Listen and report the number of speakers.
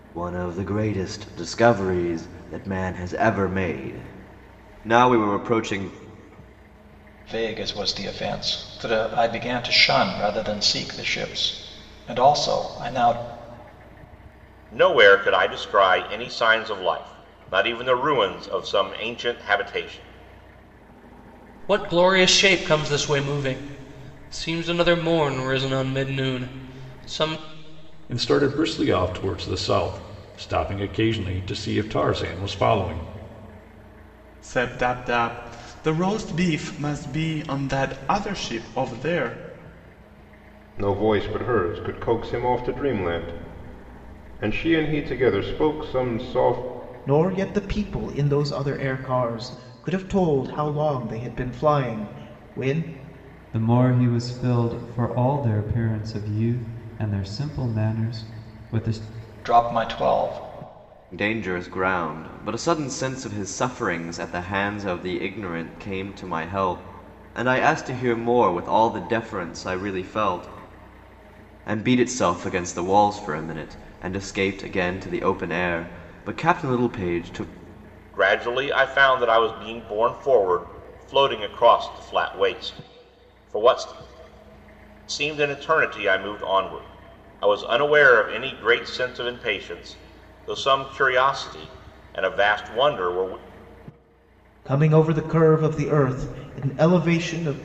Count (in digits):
9